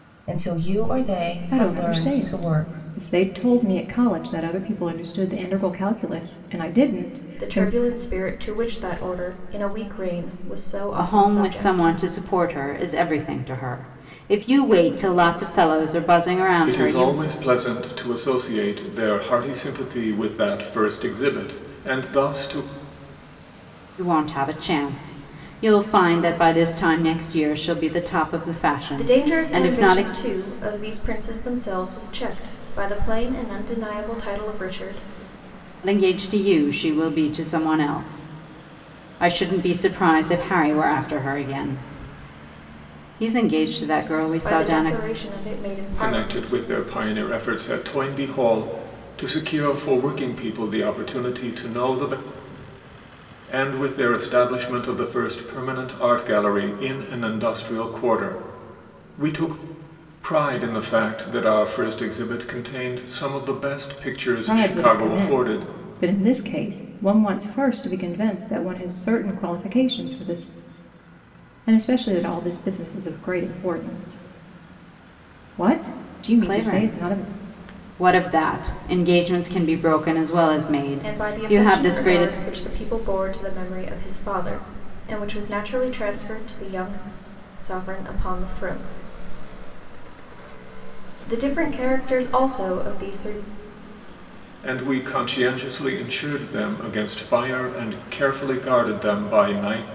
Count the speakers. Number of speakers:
five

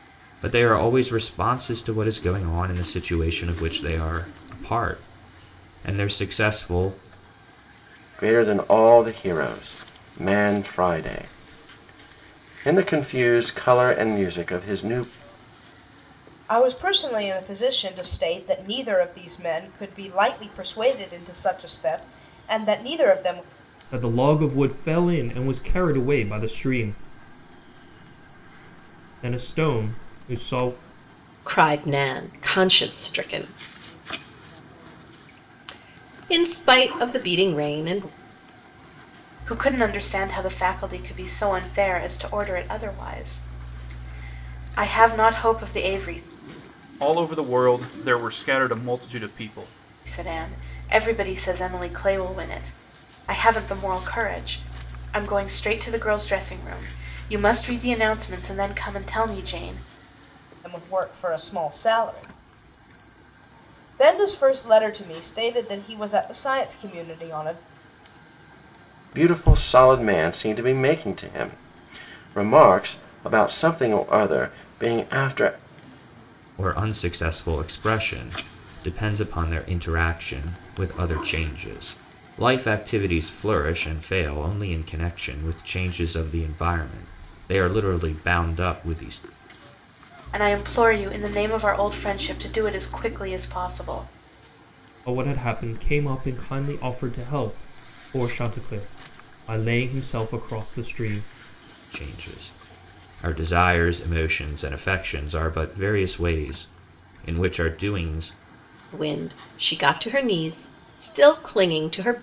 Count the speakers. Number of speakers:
seven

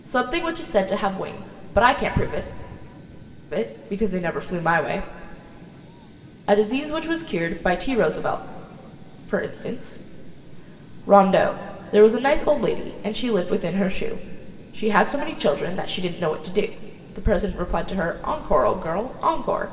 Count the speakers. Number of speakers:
one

